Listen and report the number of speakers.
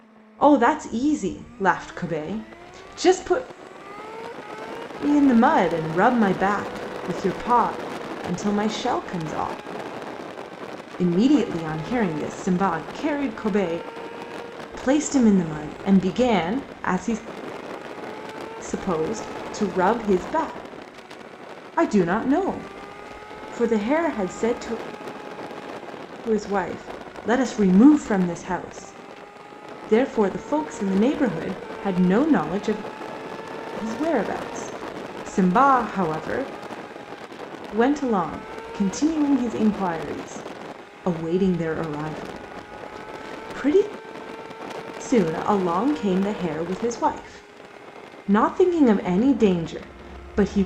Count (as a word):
one